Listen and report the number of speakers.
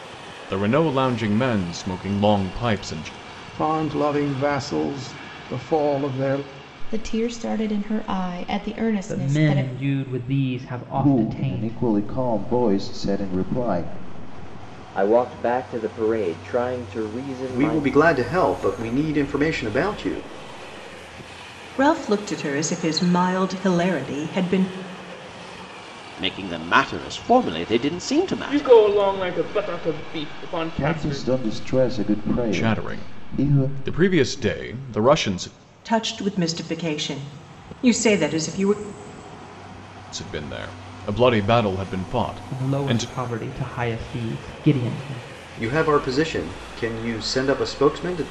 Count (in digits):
10